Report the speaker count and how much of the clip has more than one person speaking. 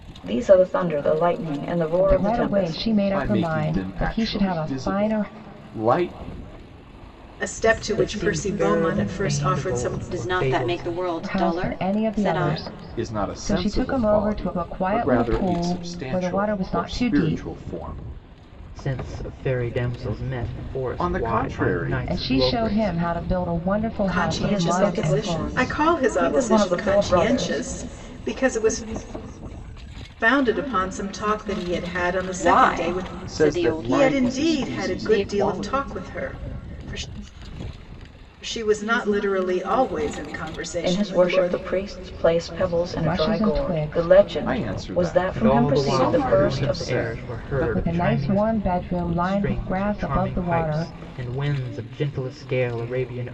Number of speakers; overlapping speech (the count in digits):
6, about 54%